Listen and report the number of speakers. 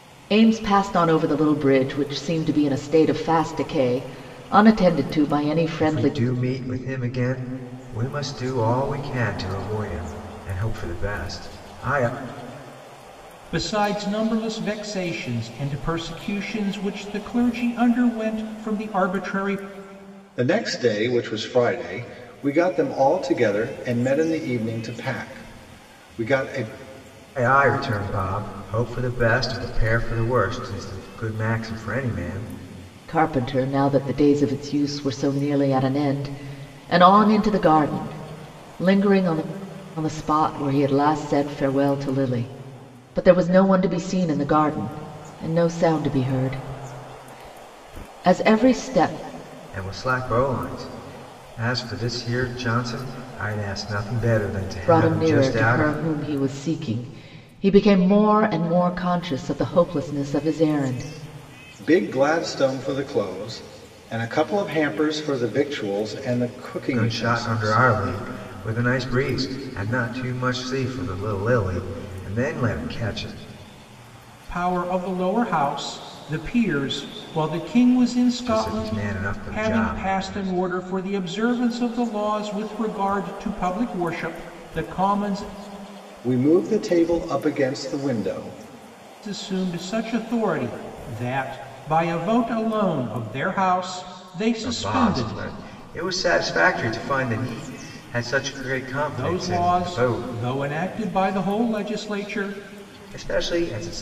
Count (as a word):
four